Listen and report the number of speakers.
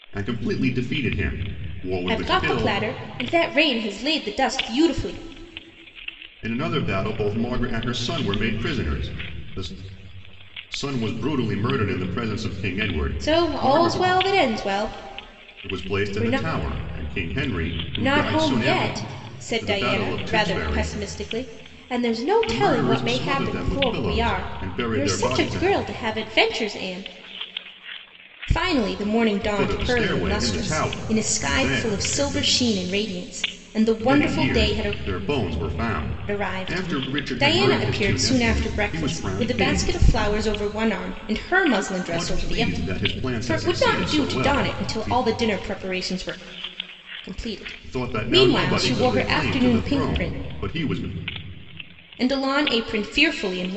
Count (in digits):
2